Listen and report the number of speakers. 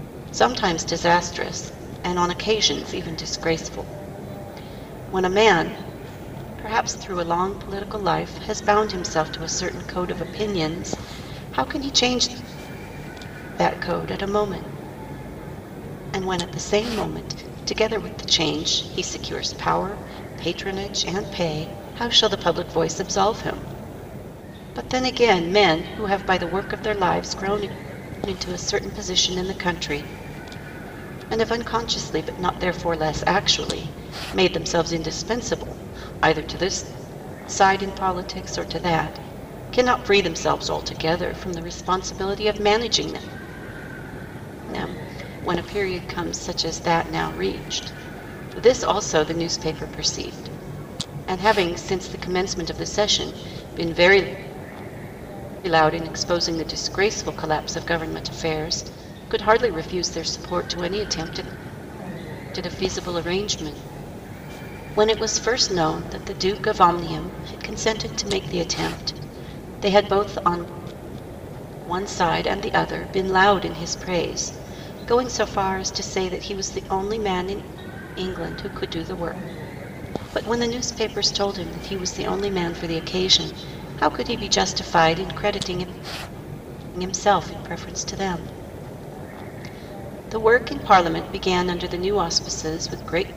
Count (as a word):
one